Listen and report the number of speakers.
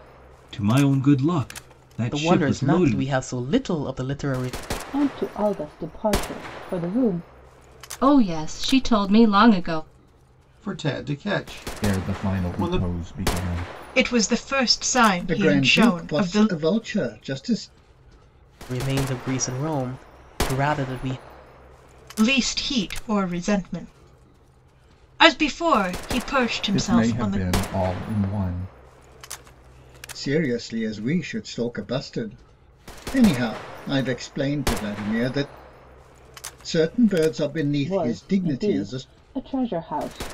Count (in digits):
8